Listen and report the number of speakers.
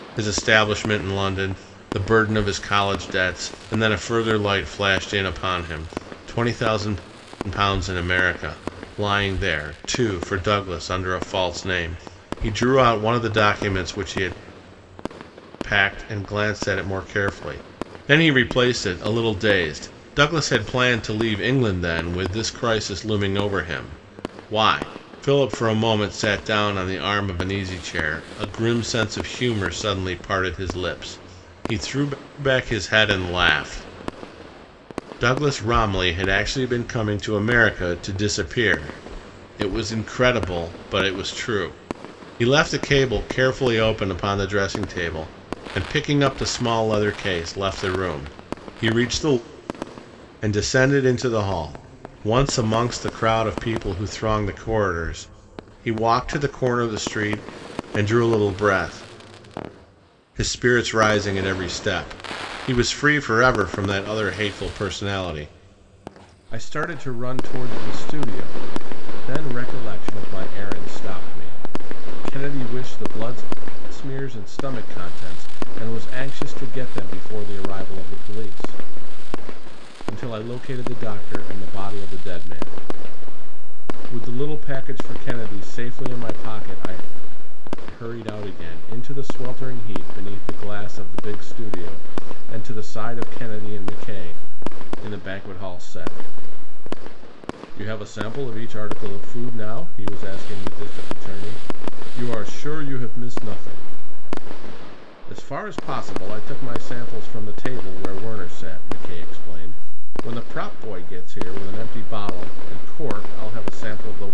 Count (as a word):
one